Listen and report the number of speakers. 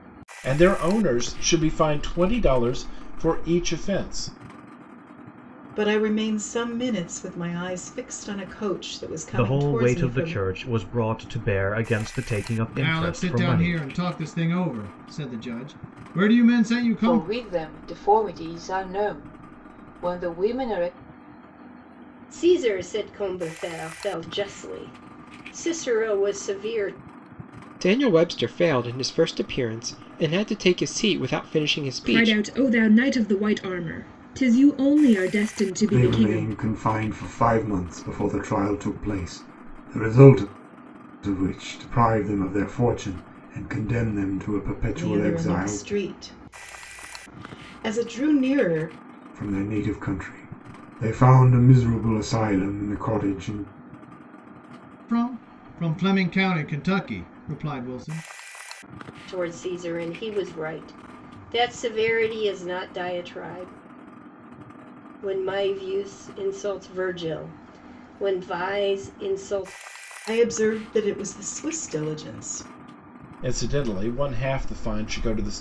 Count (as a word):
nine